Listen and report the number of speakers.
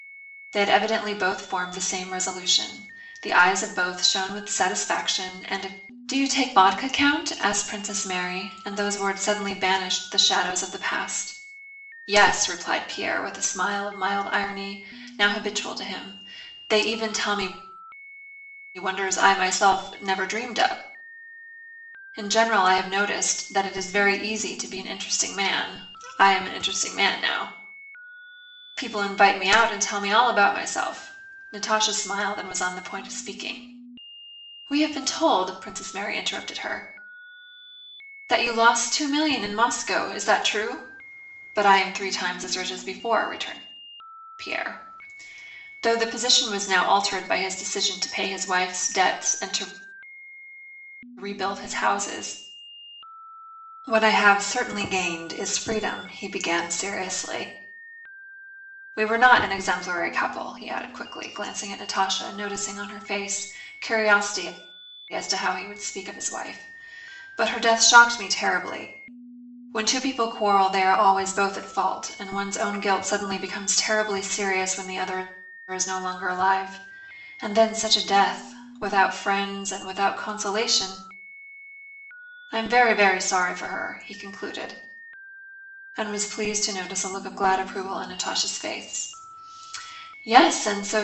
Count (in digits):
1